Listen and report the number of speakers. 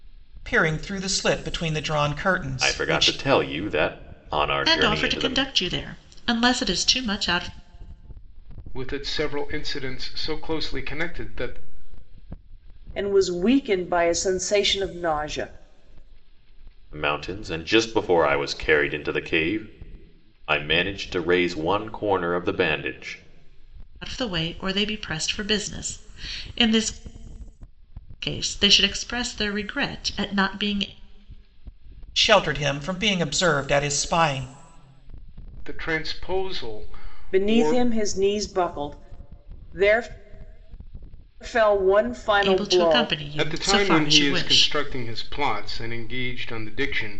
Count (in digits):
5